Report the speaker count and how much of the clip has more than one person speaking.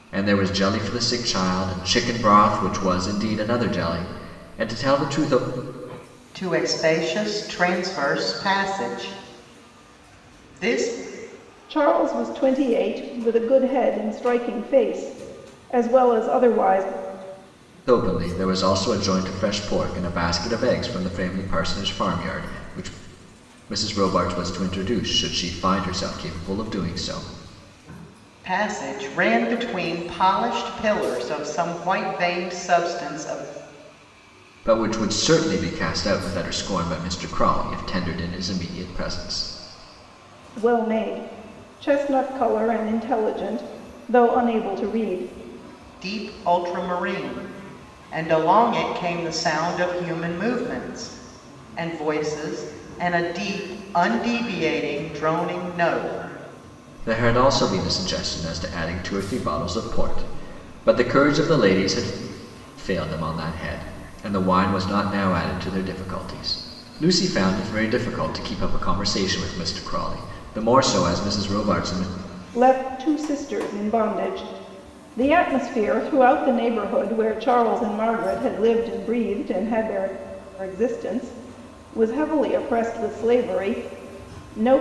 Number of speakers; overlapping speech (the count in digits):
3, no overlap